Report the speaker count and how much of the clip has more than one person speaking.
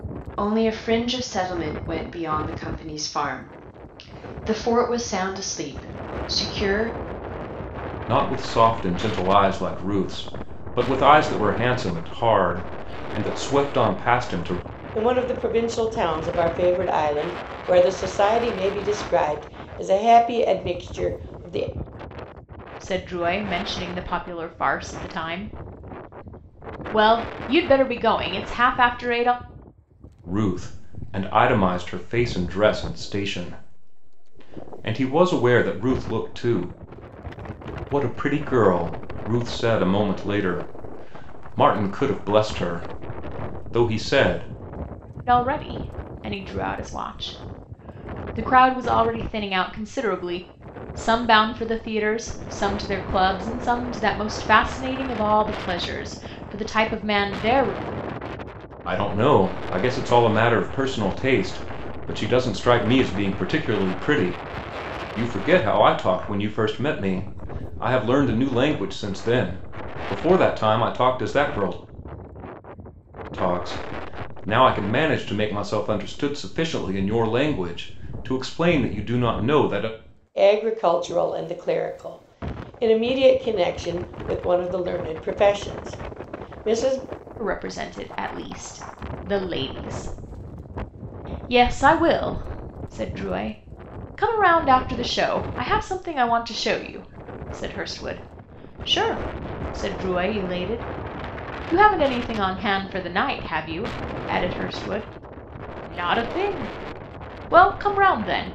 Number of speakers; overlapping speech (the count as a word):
four, no overlap